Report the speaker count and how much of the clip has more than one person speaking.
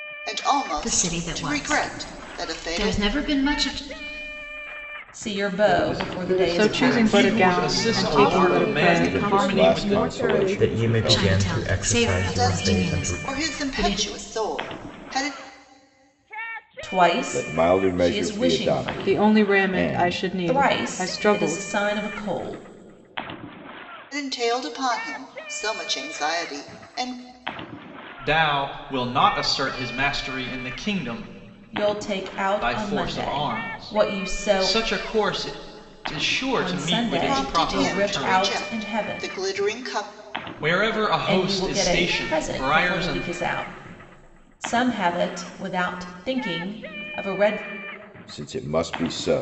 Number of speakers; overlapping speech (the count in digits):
9, about 45%